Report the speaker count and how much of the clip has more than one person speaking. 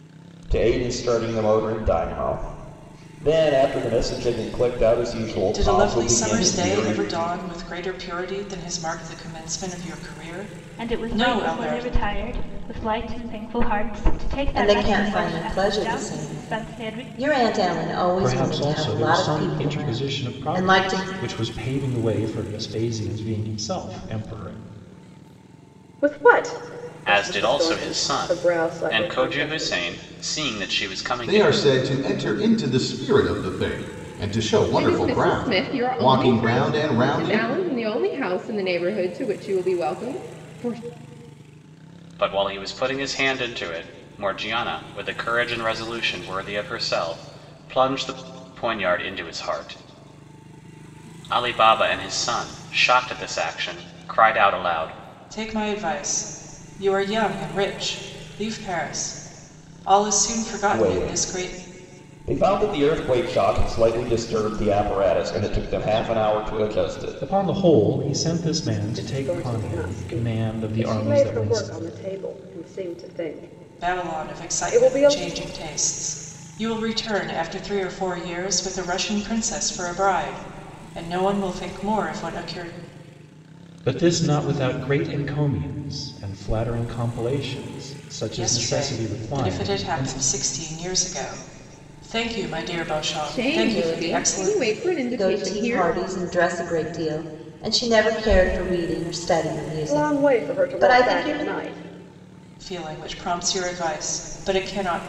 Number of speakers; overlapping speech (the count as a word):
nine, about 26%